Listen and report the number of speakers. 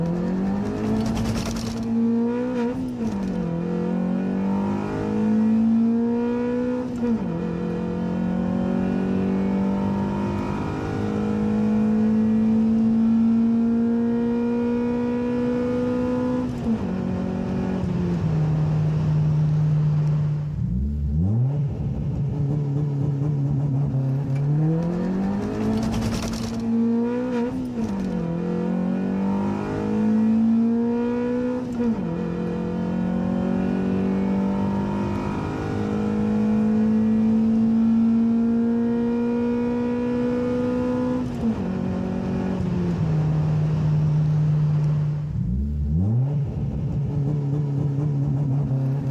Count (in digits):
0